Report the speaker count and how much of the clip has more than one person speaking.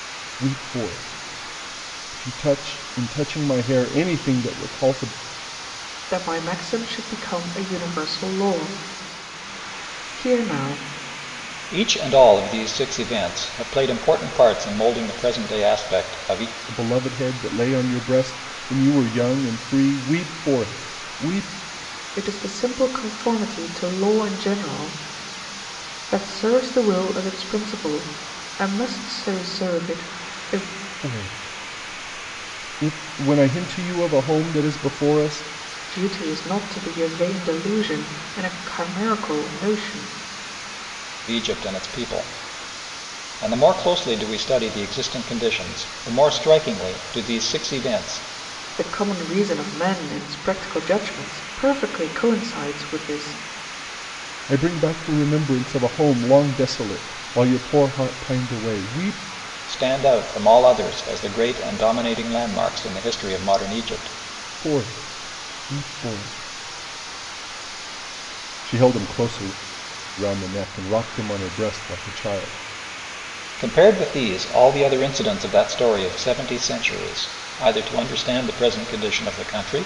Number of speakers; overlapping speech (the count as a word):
three, no overlap